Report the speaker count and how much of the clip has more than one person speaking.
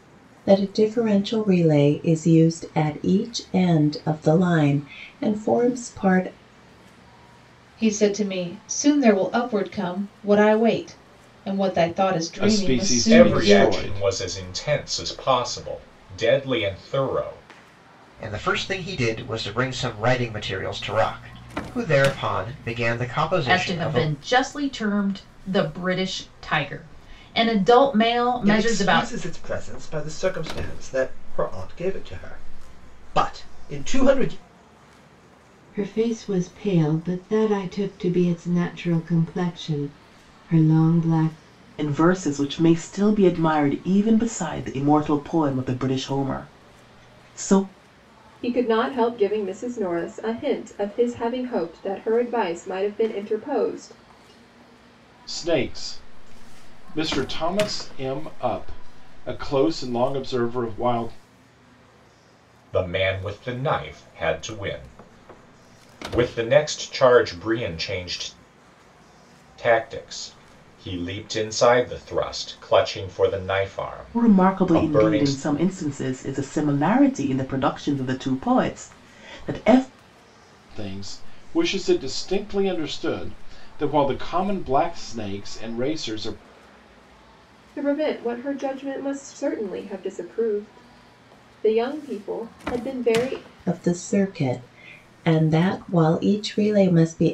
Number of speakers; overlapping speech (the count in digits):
10, about 4%